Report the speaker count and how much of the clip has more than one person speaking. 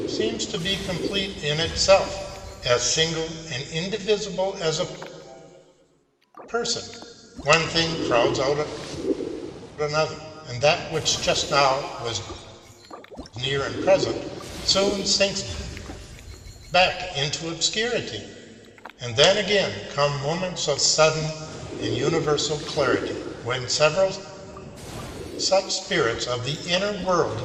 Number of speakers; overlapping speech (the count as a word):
one, no overlap